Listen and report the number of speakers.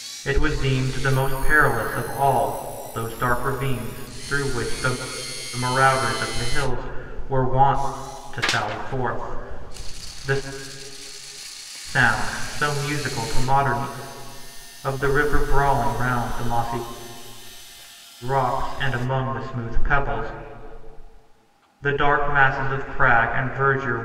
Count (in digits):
1